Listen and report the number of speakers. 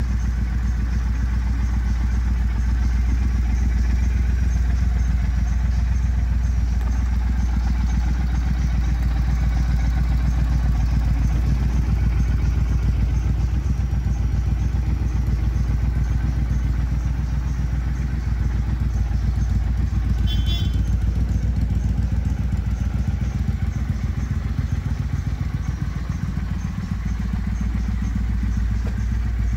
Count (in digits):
0